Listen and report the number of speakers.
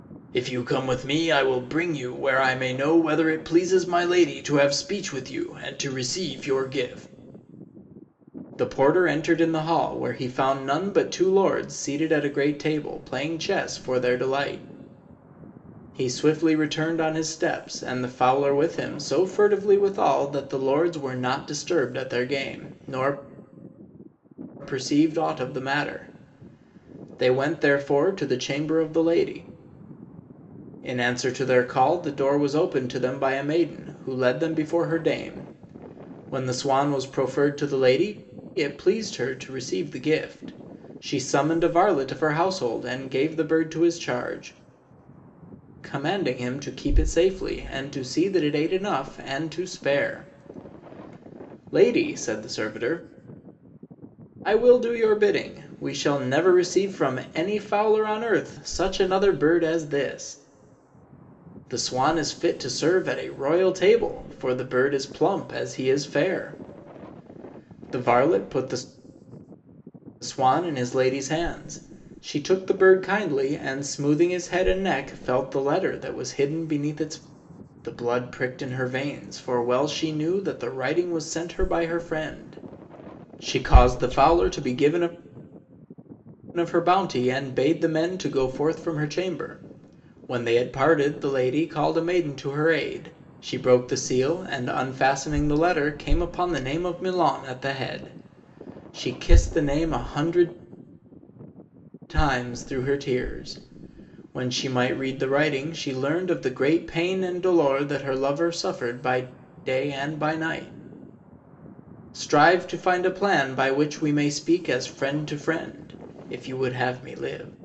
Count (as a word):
one